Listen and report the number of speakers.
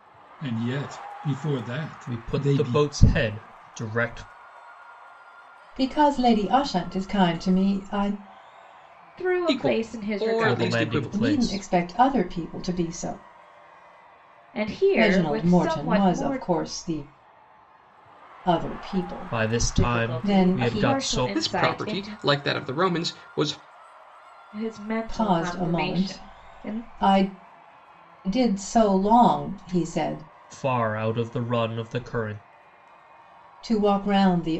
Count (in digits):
5